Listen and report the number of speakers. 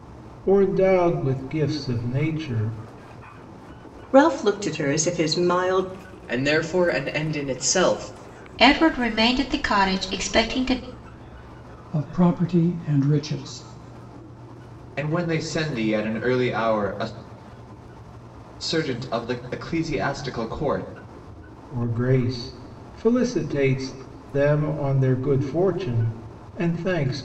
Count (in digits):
6